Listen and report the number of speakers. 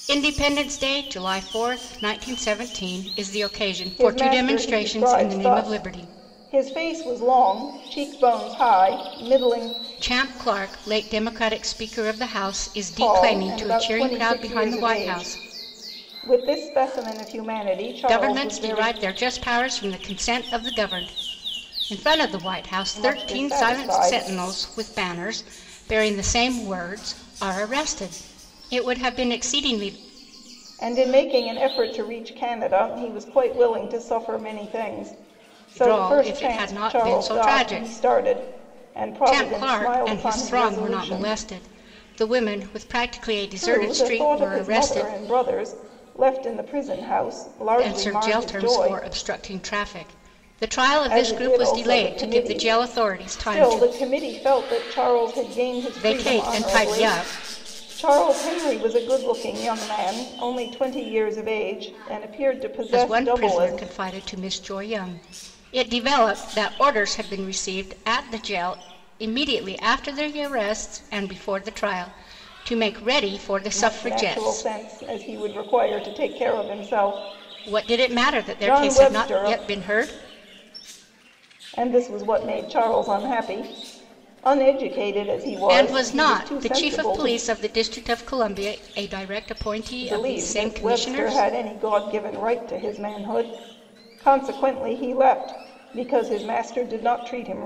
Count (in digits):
2